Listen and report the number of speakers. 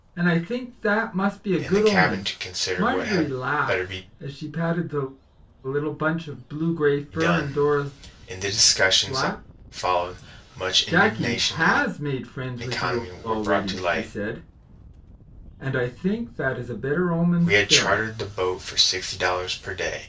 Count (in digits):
2